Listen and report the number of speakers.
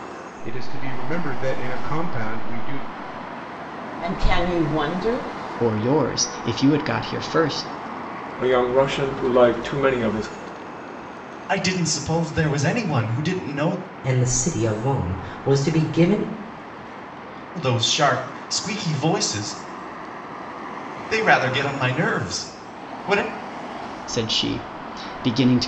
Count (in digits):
6